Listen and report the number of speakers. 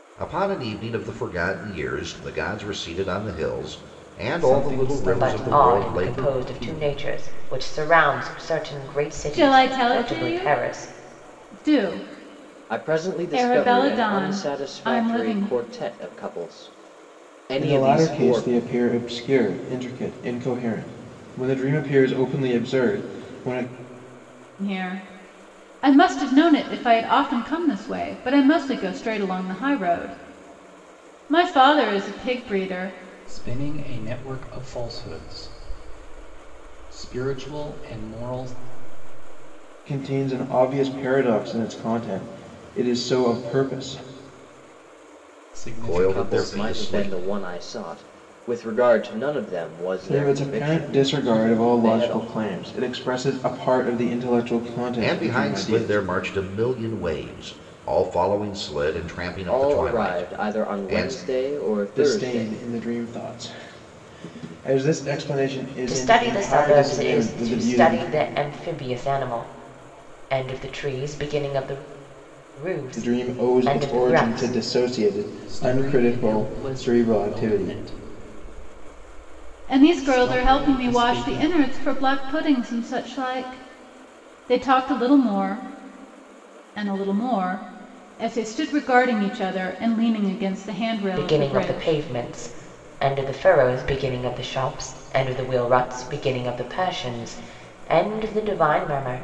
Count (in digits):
6